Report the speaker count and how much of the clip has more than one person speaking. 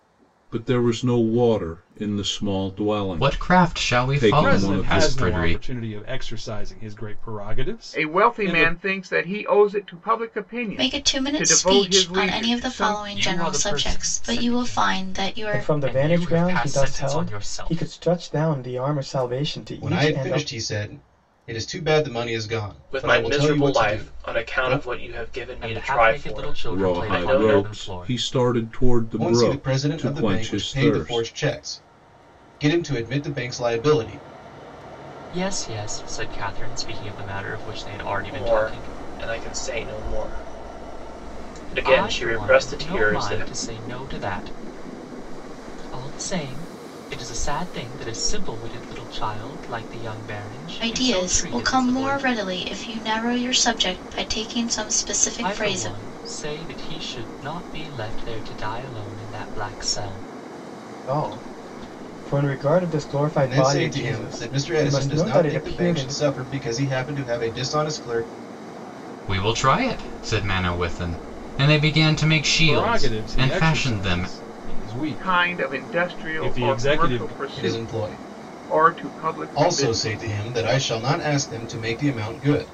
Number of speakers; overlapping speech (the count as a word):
nine, about 38%